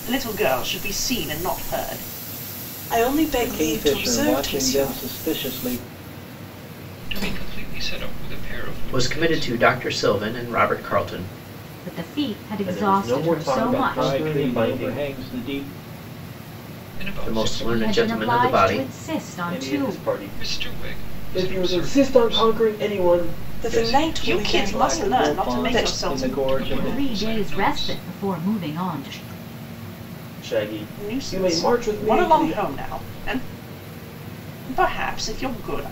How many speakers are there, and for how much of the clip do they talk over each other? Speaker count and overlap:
7, about 44%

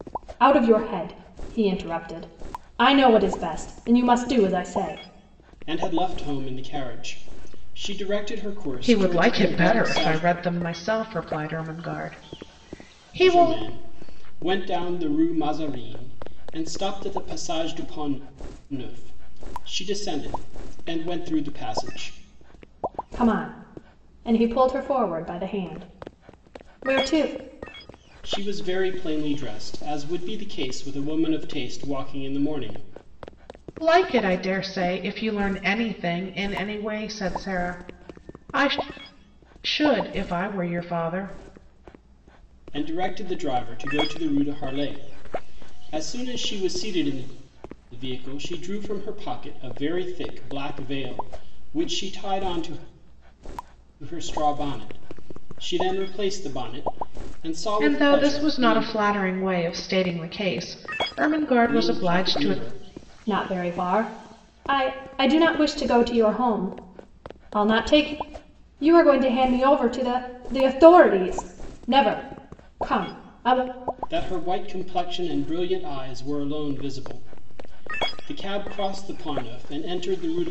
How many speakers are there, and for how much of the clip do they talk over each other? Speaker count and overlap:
3, about 5%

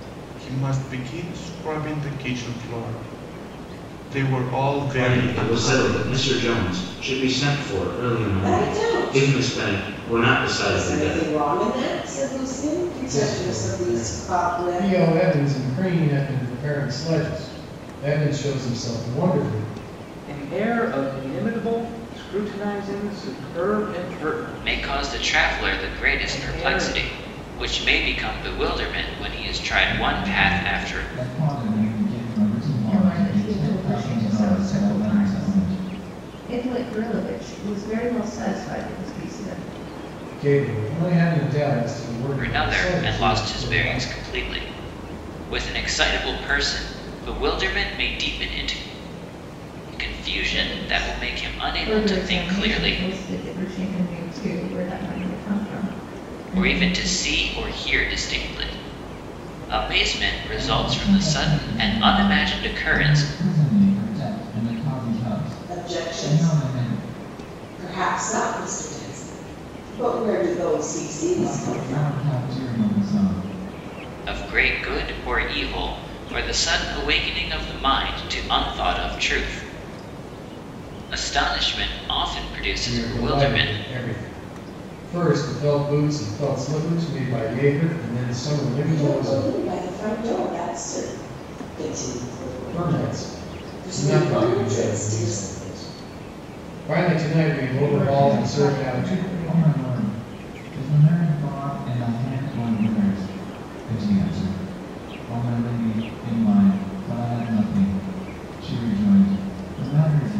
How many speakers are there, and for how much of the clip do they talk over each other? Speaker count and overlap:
9, about 27%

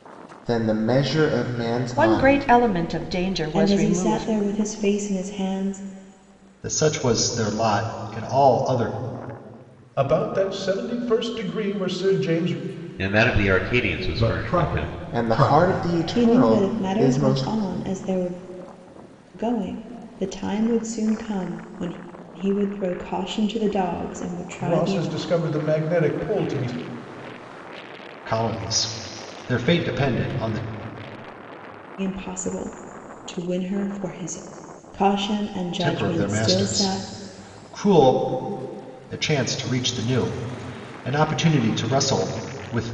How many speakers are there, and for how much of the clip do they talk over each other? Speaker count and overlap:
7, about 15%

